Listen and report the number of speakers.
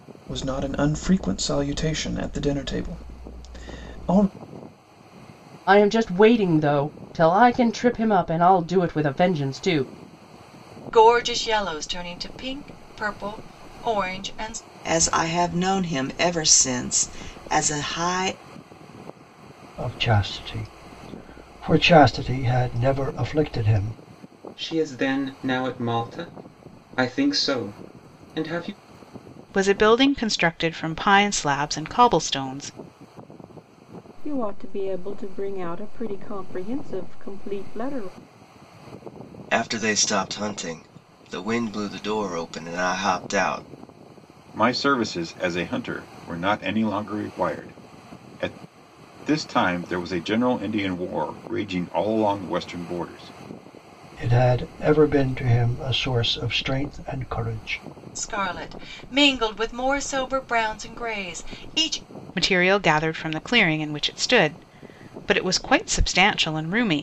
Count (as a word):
ten